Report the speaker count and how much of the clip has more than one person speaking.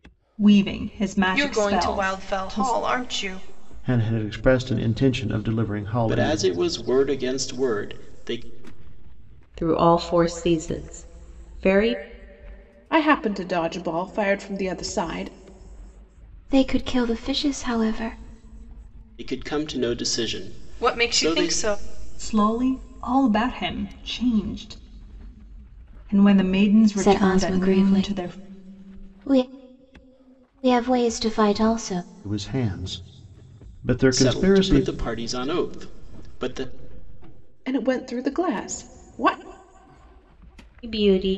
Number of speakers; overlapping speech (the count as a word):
seven, about 12%